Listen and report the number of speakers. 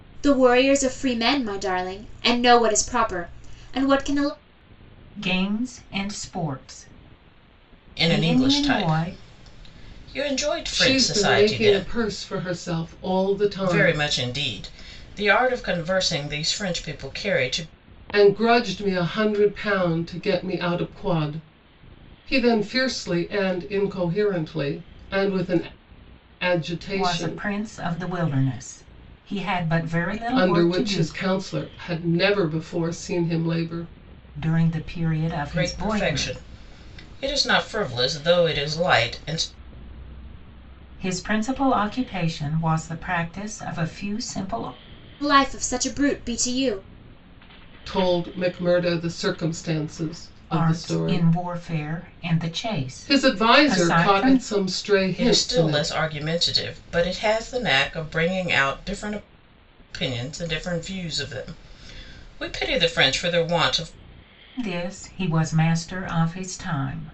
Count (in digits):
4